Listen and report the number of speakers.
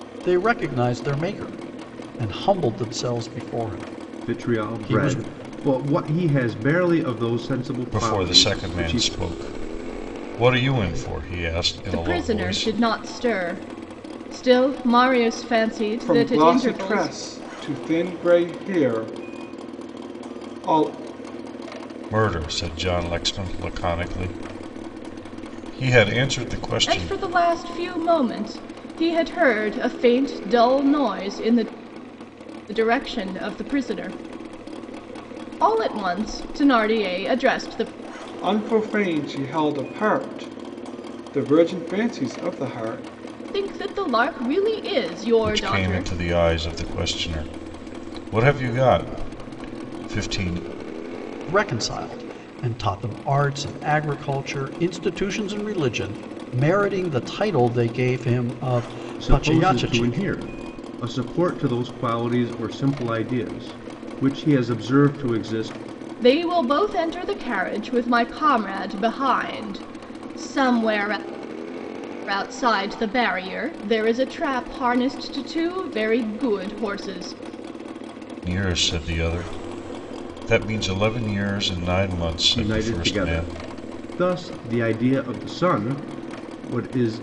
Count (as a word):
five